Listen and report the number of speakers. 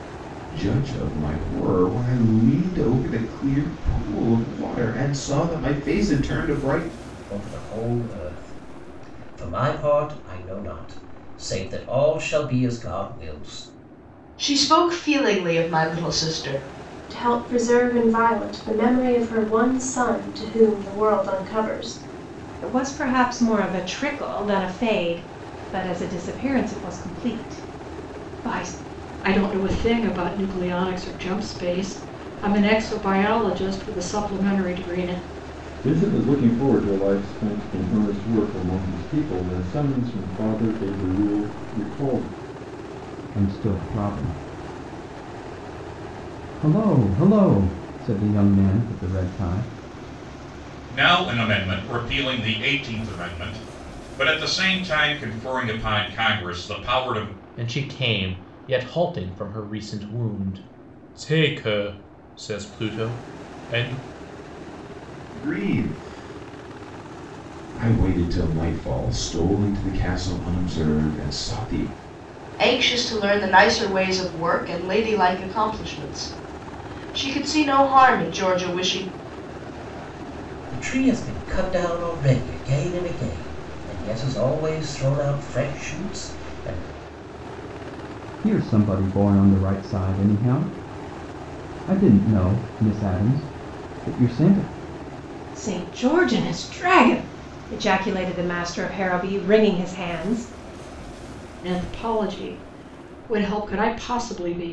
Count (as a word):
ten